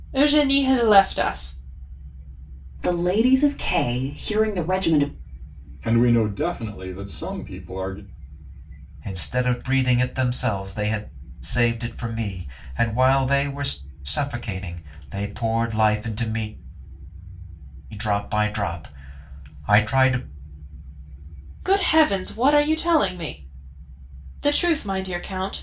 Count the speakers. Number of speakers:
4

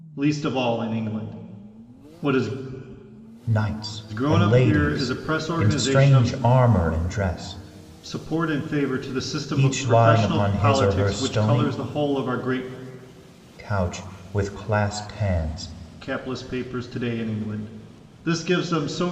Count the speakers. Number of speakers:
2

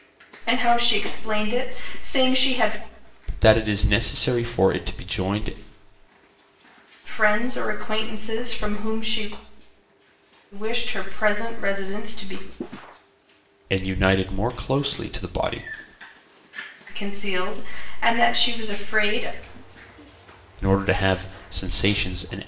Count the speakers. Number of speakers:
2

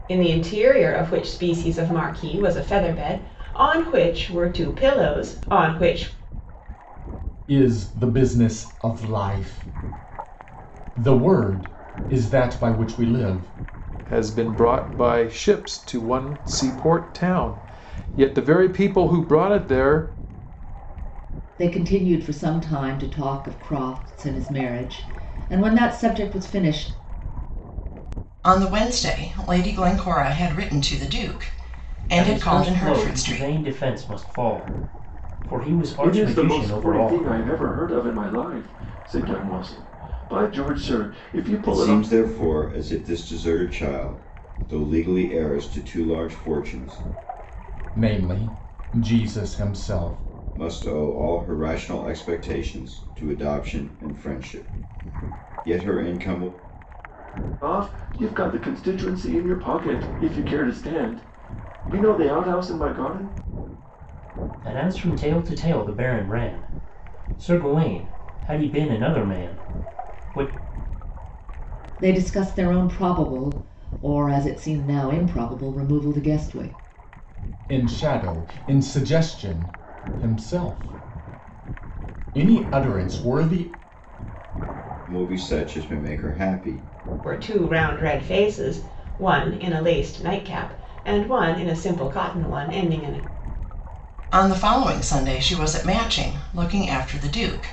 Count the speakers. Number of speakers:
8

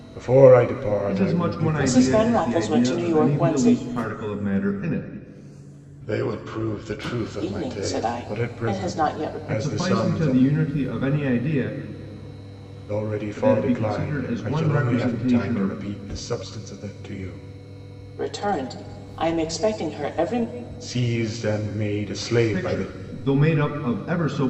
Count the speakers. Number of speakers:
3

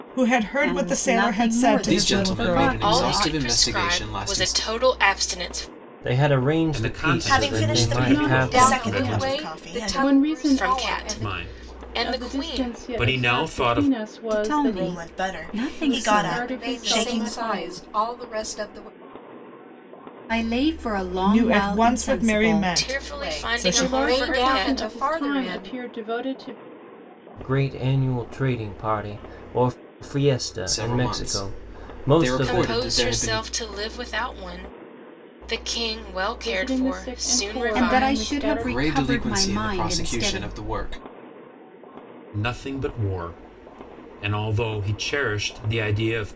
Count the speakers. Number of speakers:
9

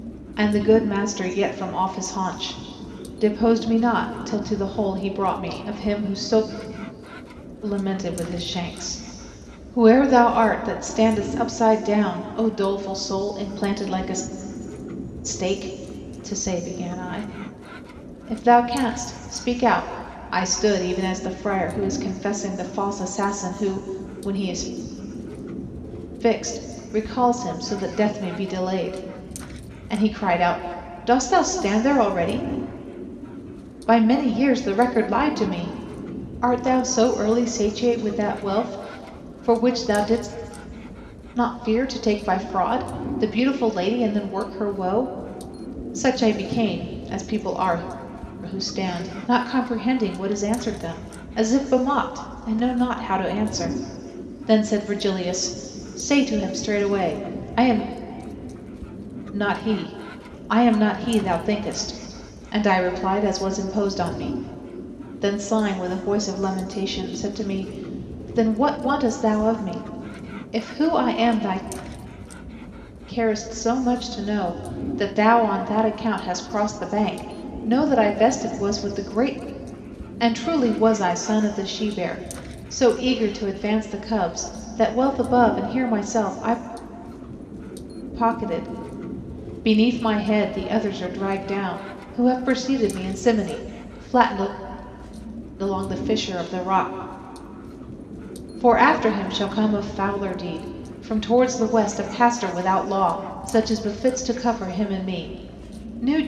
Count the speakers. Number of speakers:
1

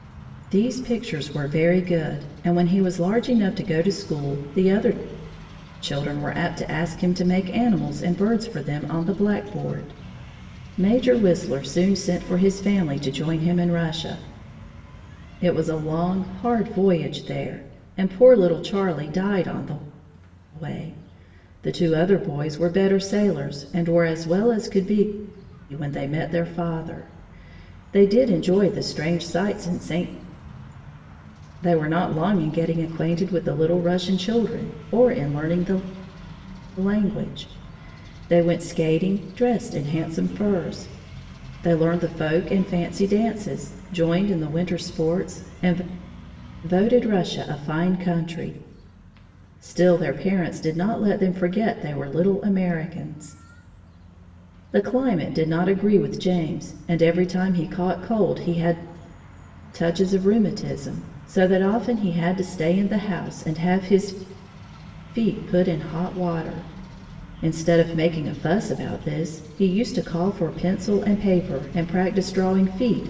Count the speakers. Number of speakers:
1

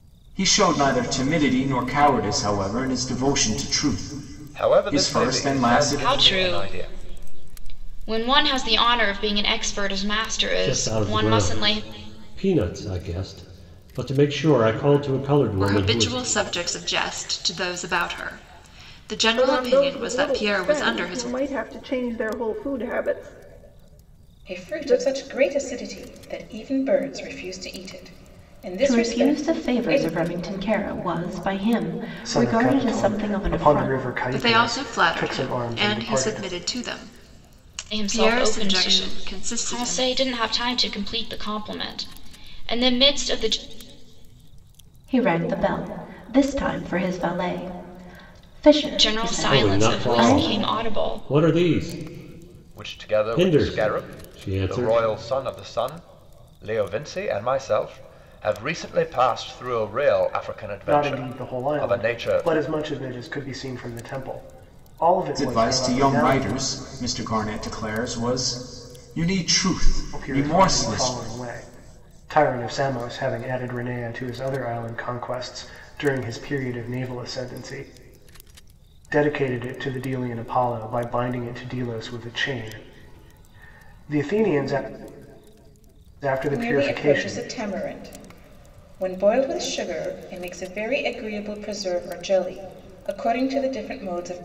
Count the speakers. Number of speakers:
9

